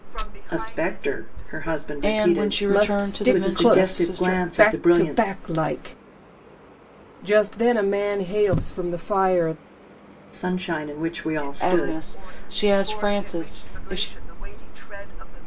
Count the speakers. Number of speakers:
four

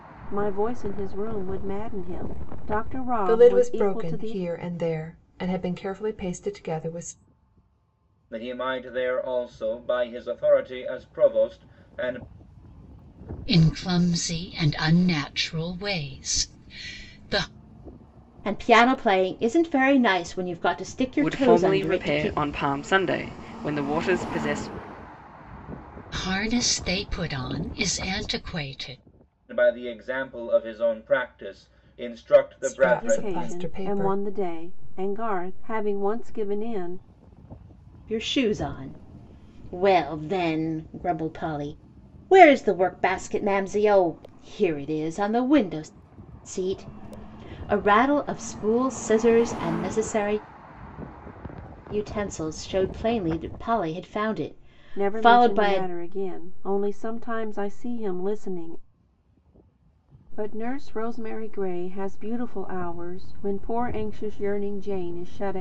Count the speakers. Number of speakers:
six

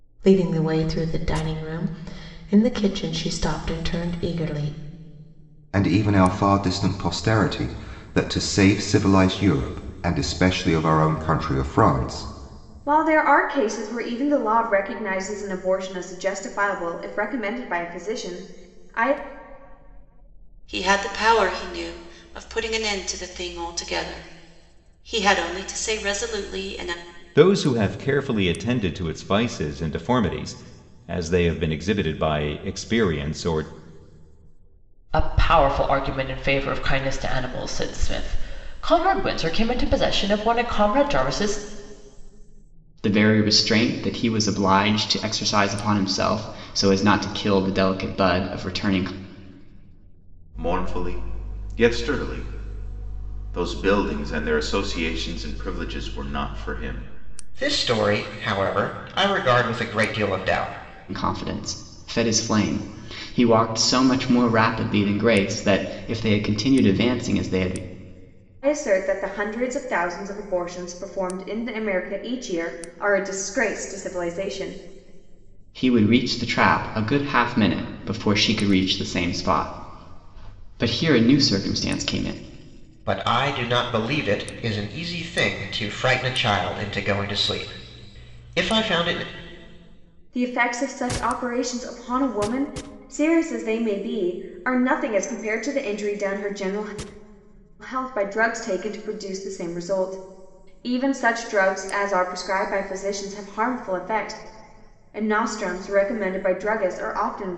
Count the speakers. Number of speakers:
nine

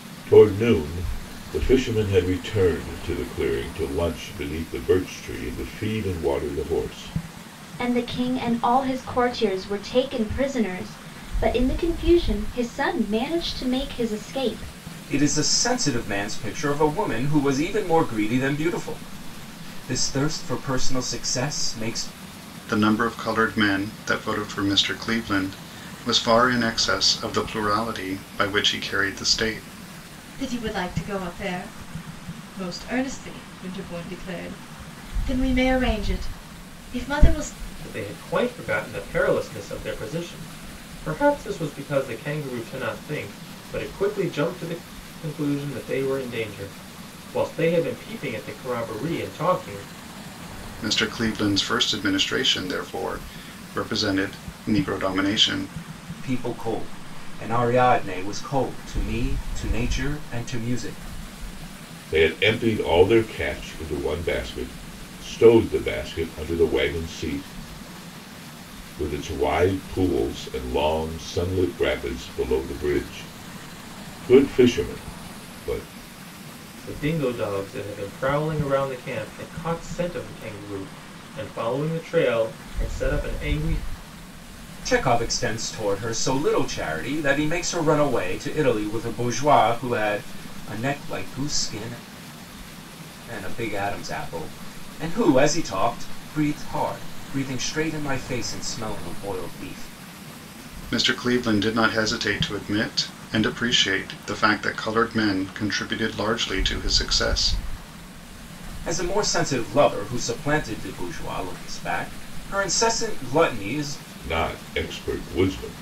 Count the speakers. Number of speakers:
six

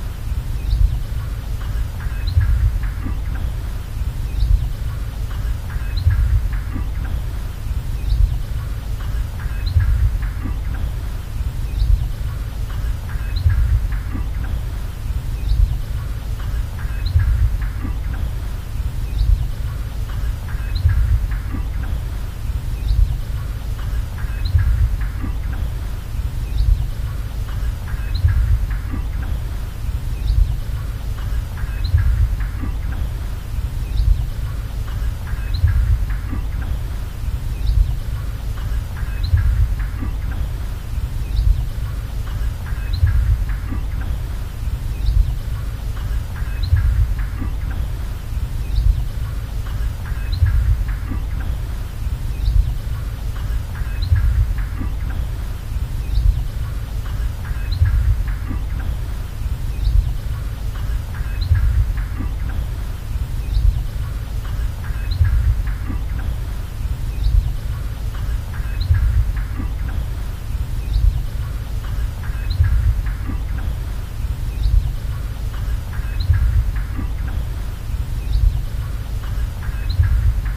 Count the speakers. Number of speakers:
zero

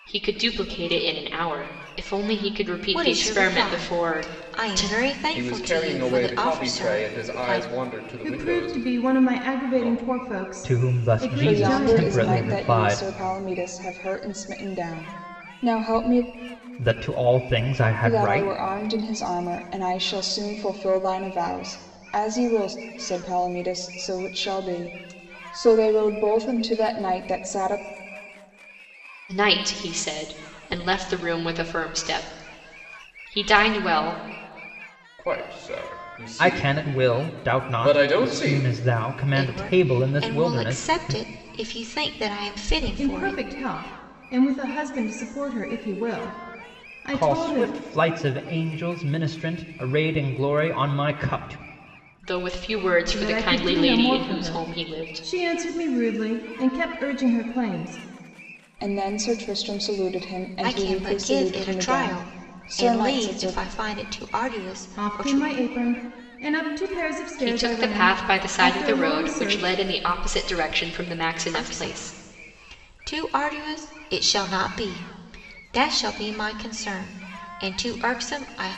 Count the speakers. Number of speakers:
six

